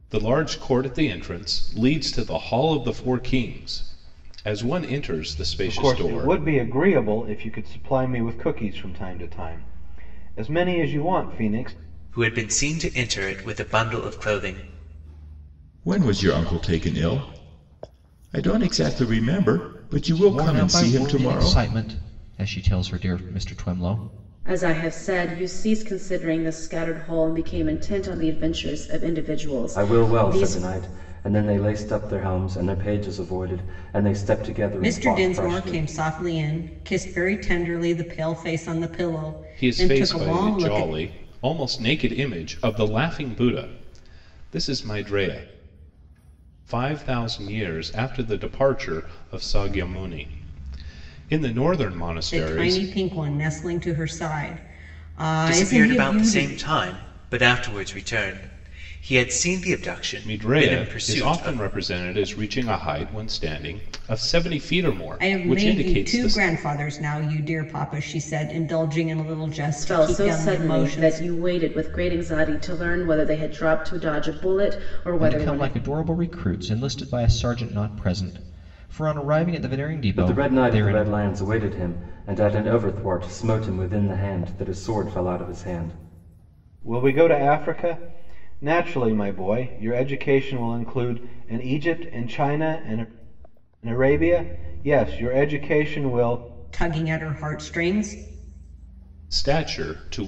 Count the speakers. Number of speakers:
8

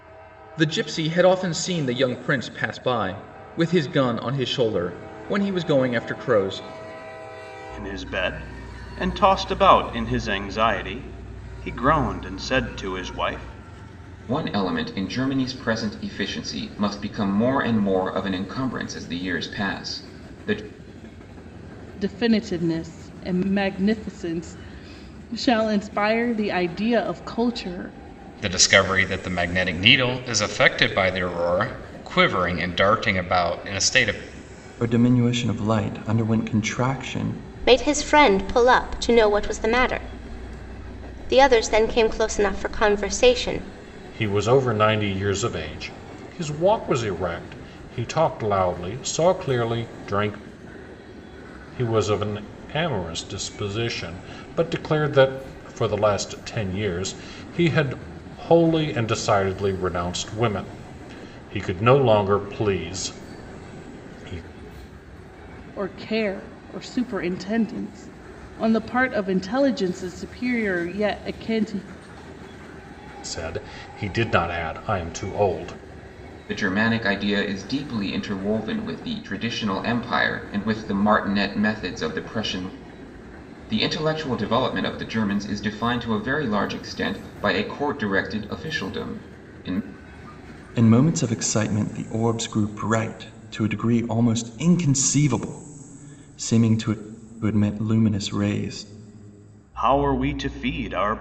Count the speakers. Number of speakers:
8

